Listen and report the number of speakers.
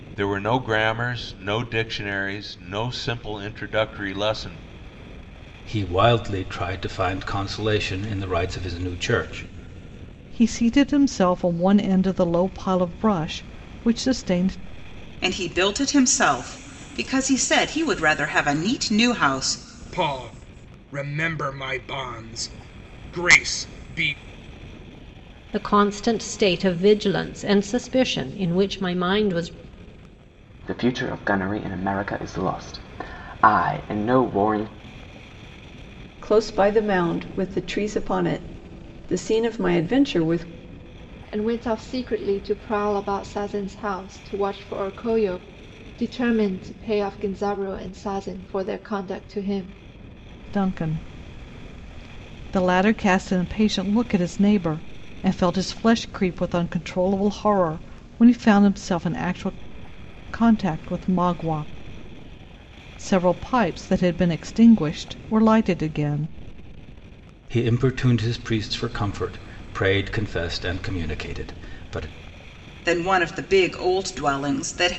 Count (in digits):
9